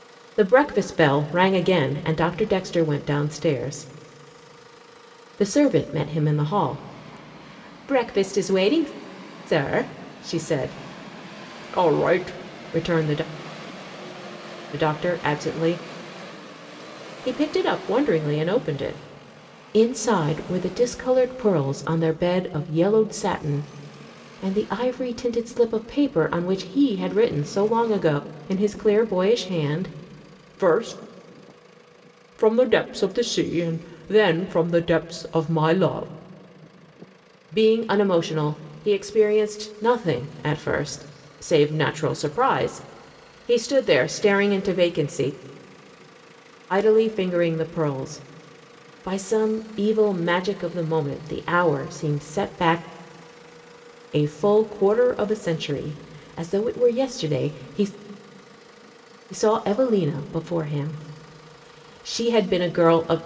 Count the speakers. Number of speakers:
1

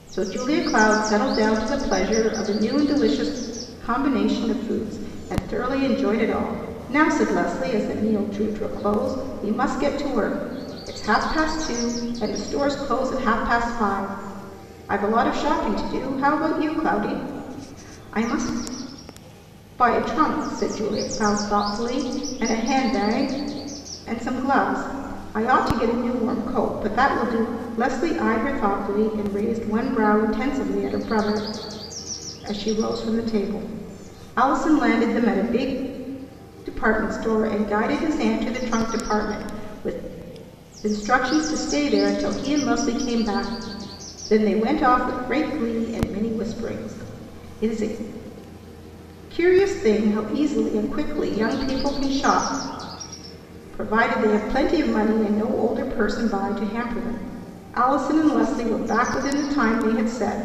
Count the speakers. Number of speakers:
1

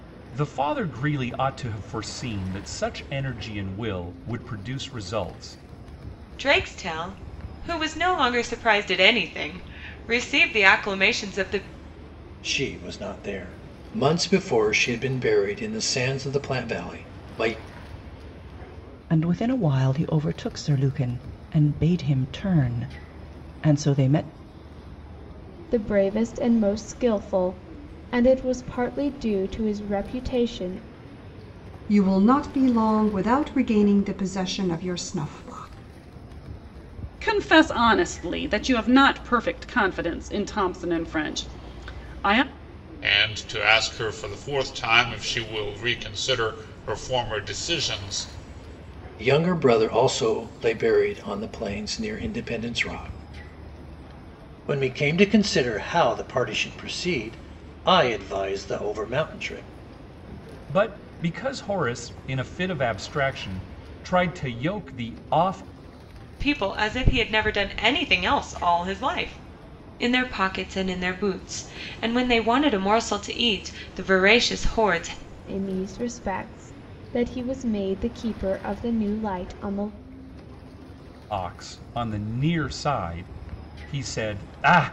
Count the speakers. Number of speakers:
8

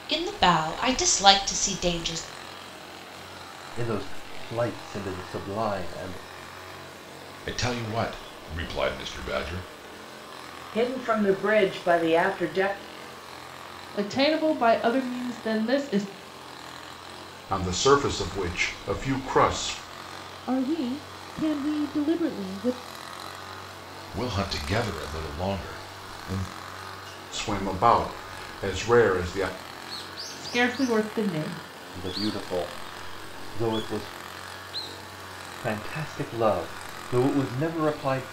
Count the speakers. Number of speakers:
7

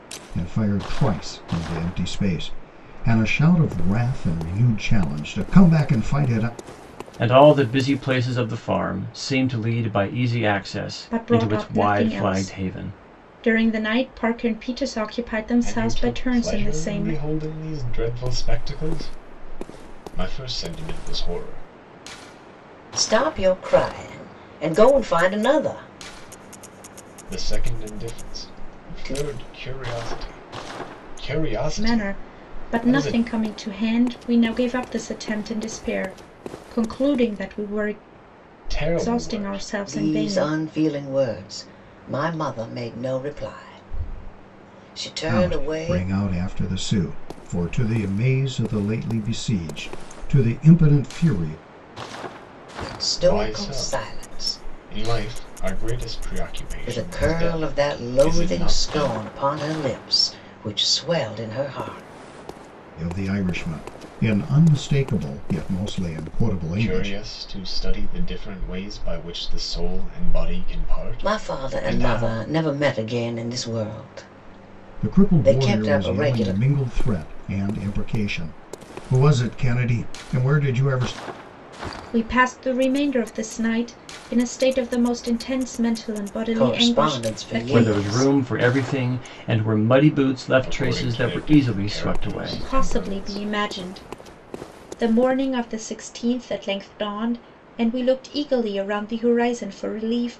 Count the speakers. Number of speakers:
5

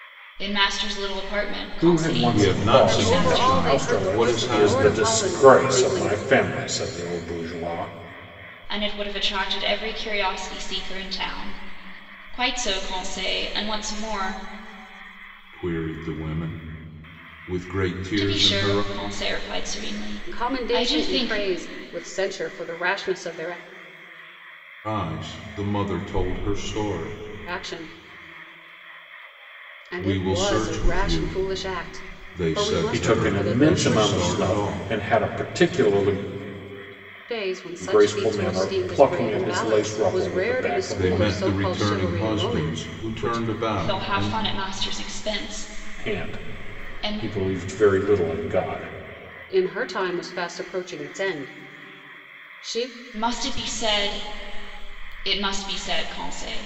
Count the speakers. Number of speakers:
4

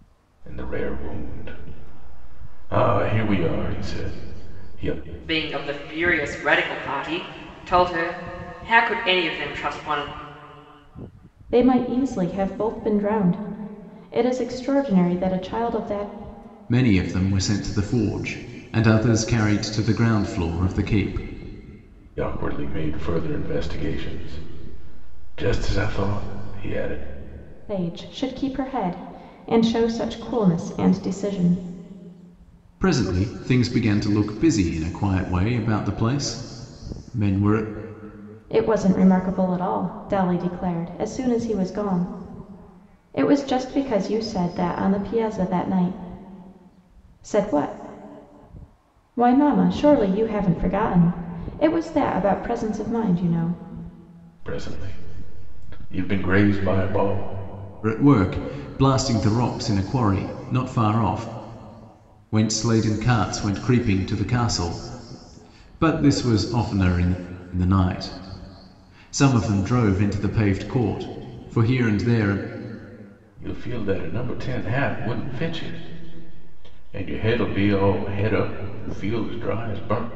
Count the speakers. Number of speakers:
4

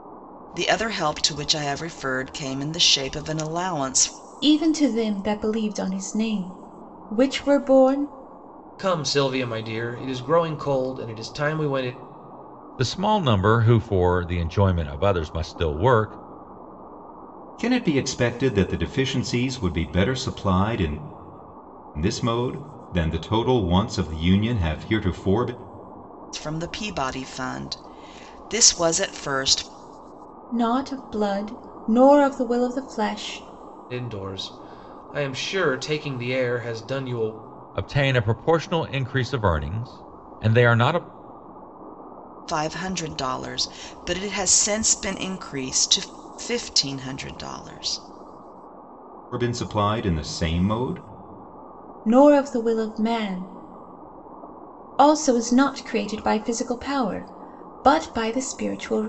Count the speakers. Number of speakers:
5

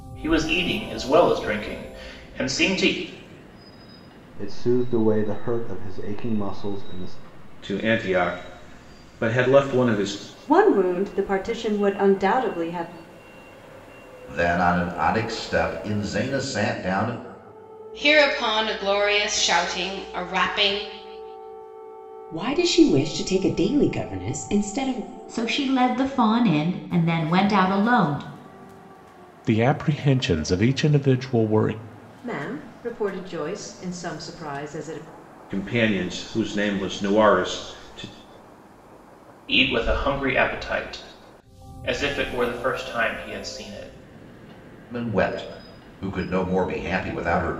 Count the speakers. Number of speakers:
10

